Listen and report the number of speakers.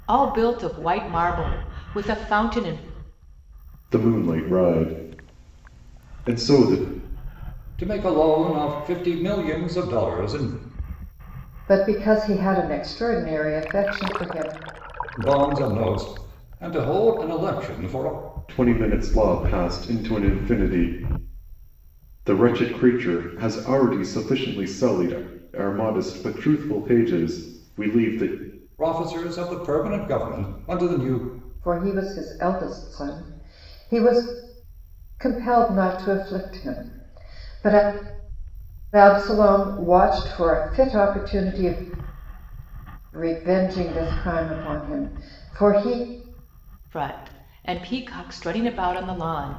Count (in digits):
4